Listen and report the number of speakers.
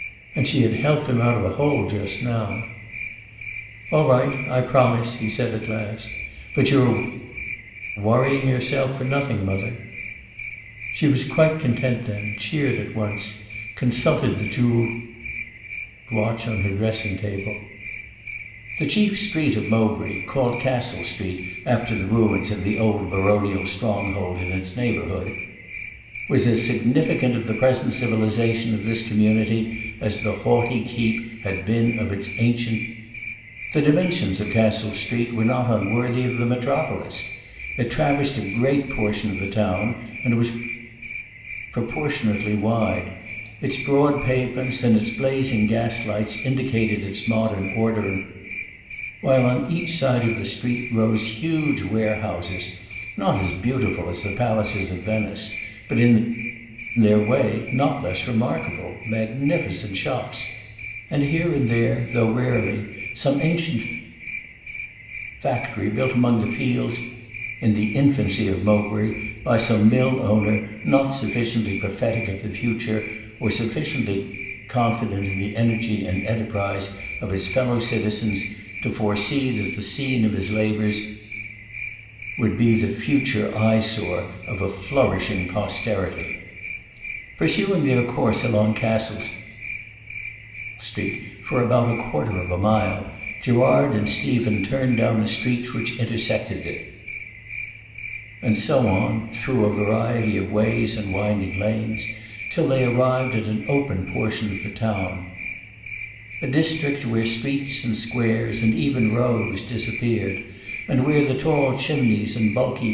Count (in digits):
1